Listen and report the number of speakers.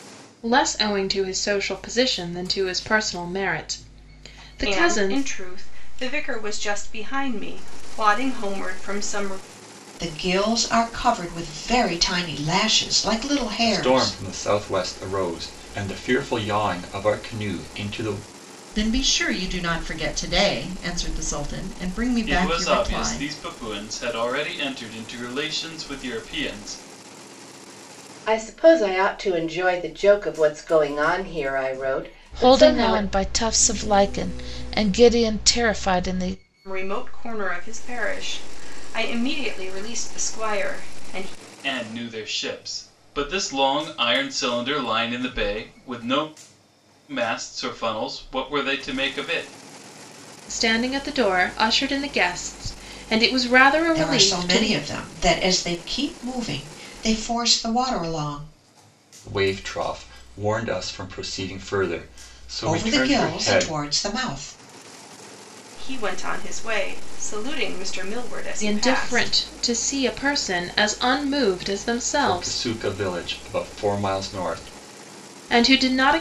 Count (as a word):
eight